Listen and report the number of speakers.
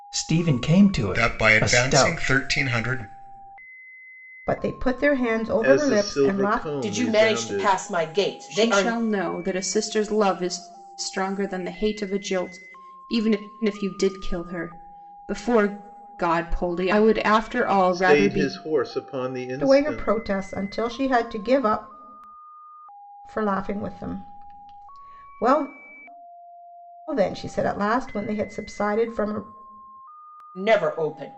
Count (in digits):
6